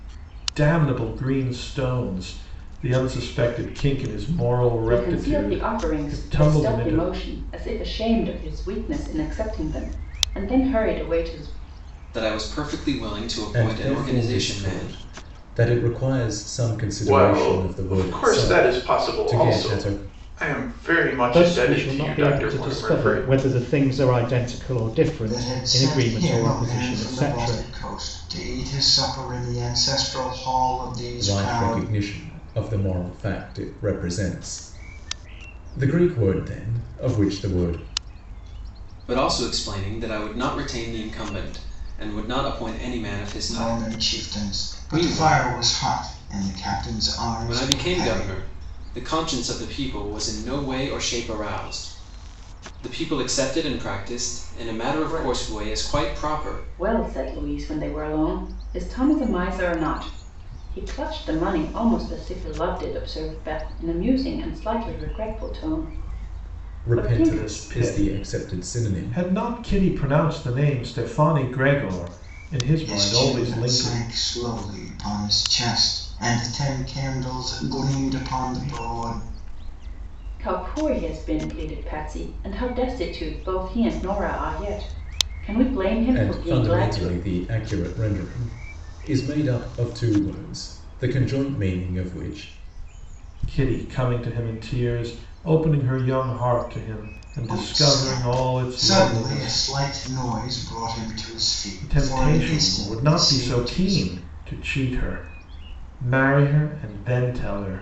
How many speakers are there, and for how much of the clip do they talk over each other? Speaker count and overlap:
7, about 24%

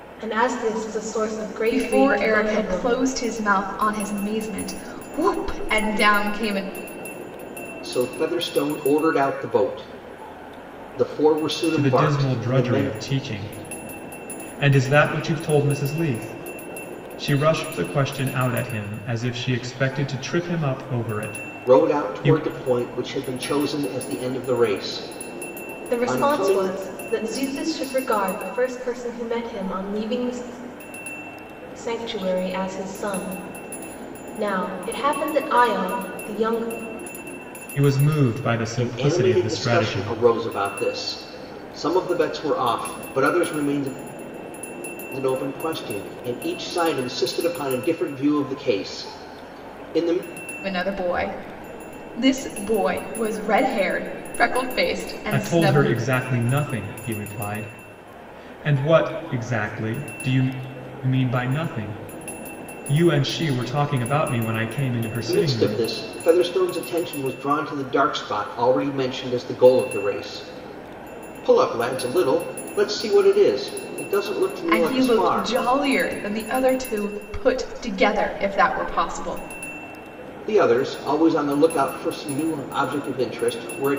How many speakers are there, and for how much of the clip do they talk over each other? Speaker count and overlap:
4, about 9%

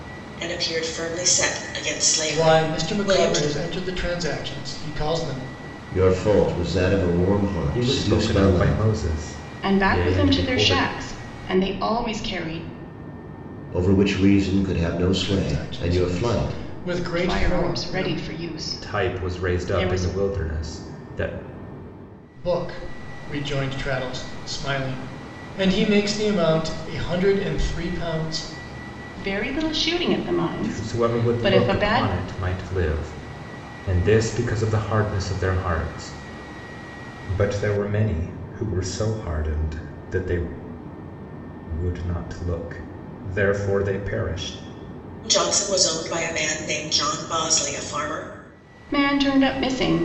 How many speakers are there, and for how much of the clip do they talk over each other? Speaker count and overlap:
5, about 18%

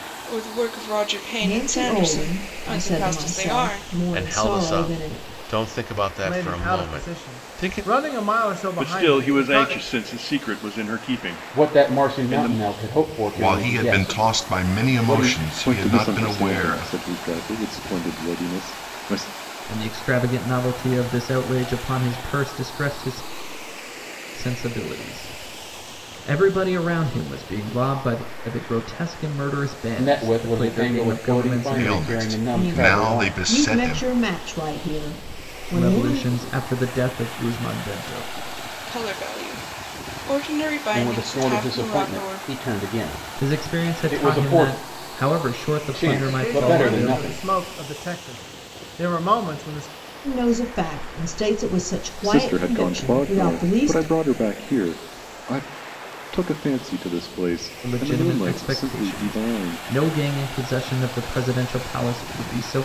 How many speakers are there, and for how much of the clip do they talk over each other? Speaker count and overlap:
9, about 38%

